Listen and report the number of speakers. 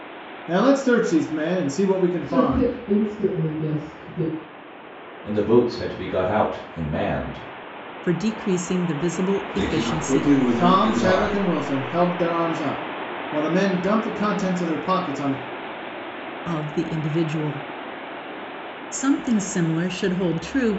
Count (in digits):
5